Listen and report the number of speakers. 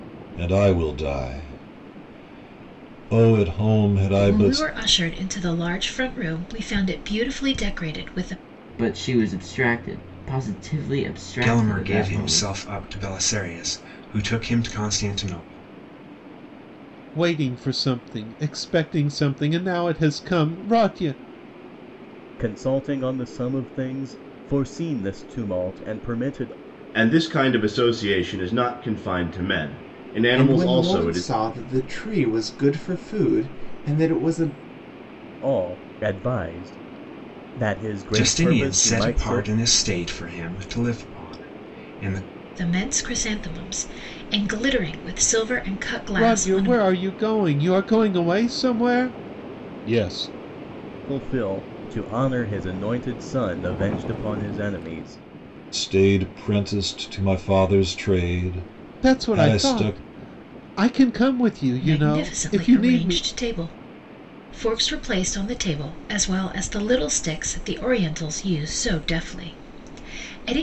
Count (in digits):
8